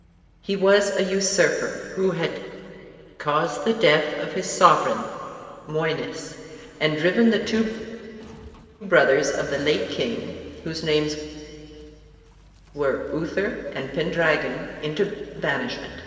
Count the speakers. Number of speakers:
1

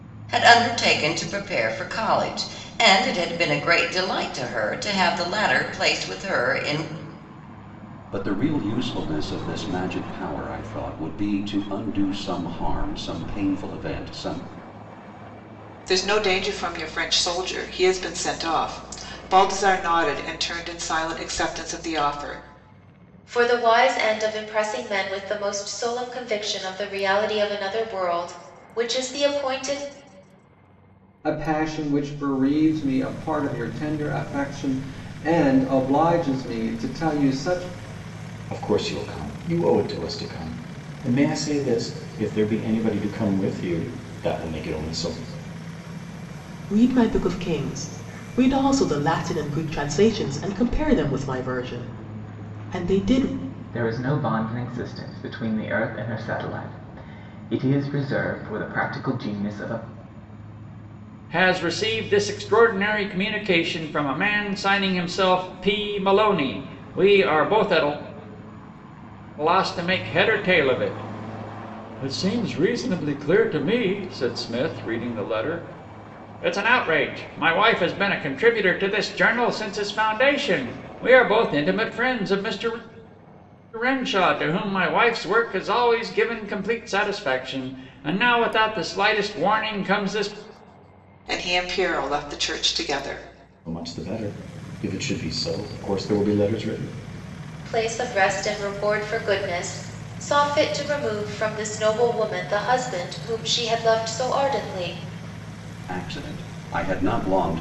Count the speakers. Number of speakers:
9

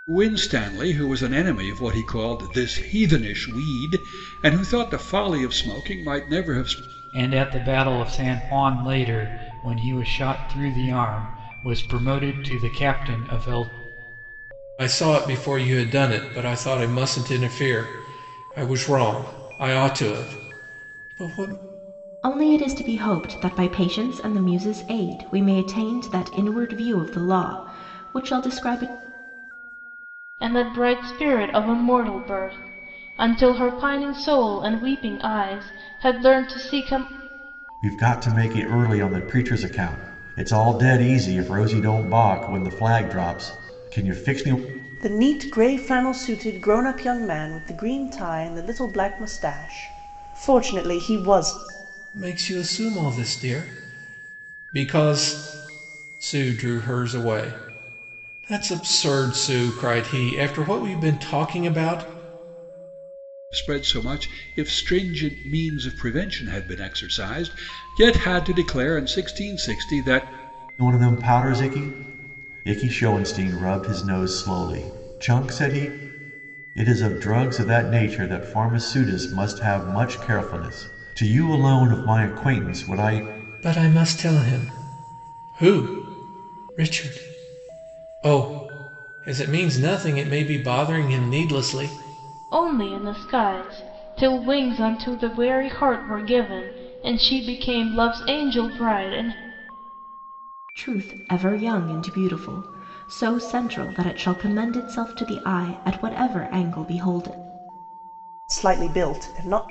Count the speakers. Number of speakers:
7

